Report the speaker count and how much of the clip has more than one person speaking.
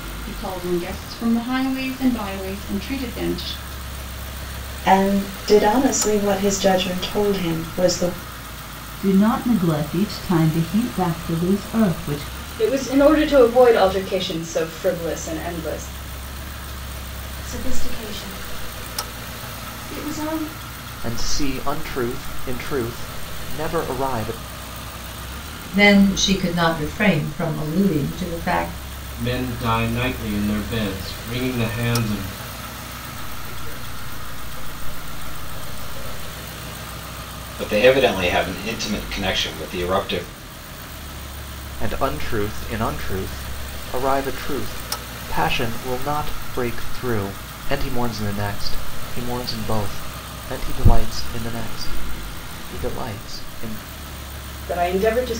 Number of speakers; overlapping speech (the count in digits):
10, no overlap